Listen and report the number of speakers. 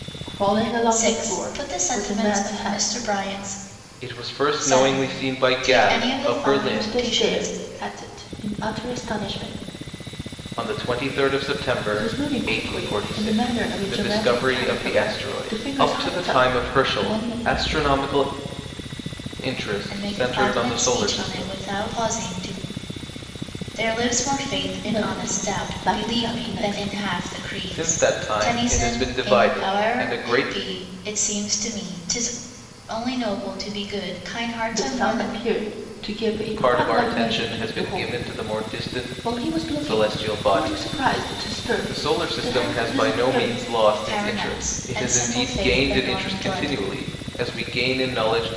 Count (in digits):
3